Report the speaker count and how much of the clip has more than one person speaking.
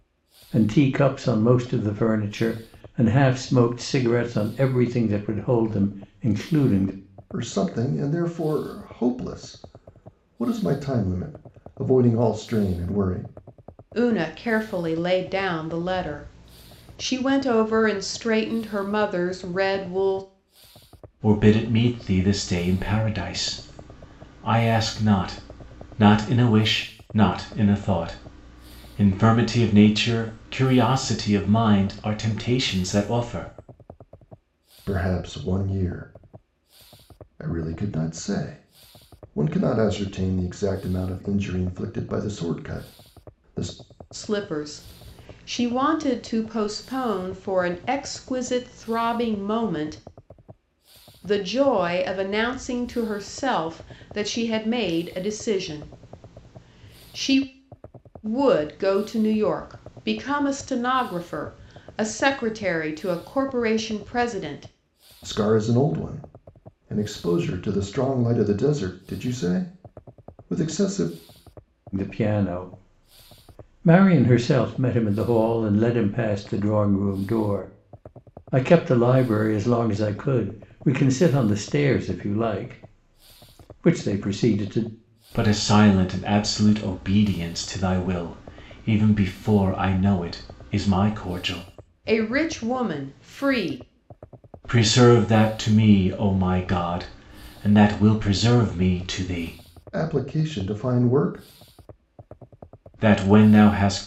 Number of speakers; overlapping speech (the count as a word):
four, no overlap